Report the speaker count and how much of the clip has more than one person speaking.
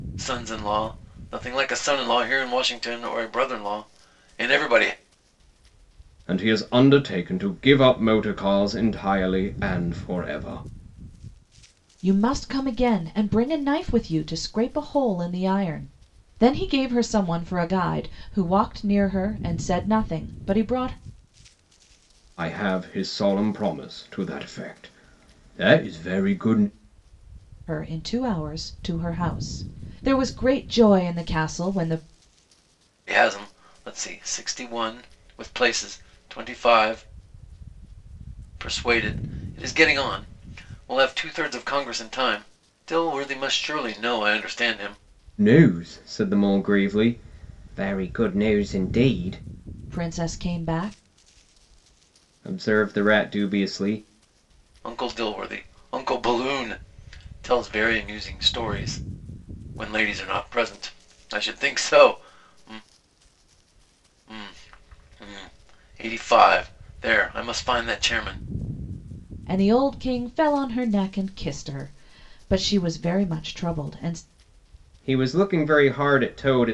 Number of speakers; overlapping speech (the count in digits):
3, no overlap